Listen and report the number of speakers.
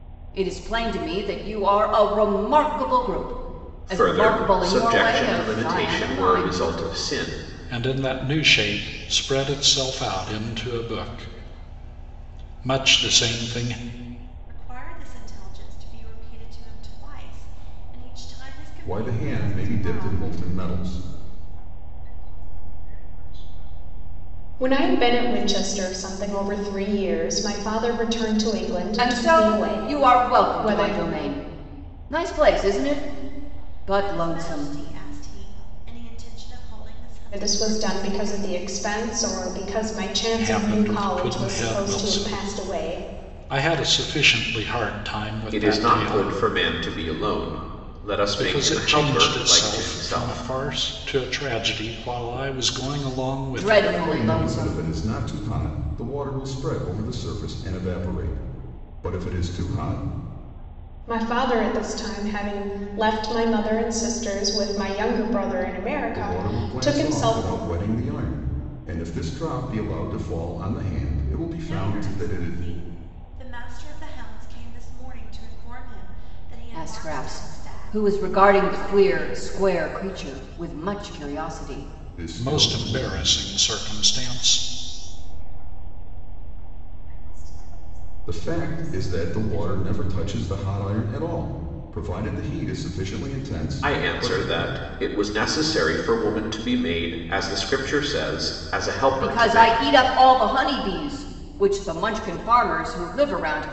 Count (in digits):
7